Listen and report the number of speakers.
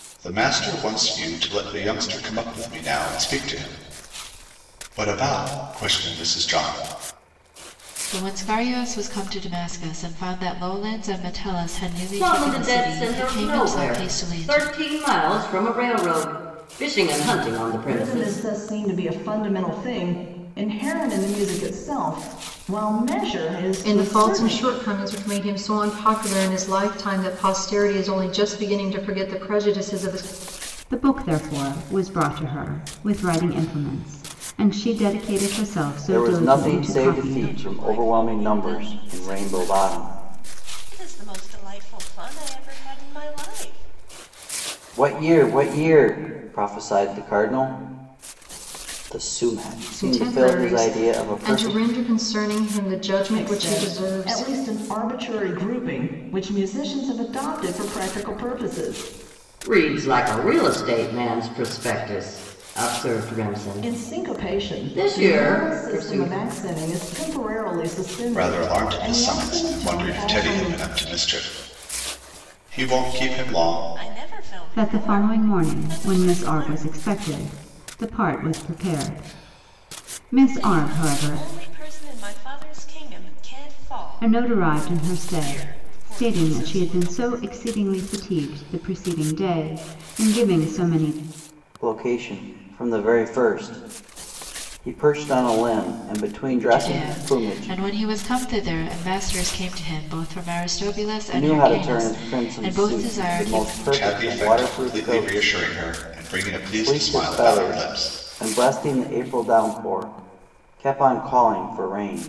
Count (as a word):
eight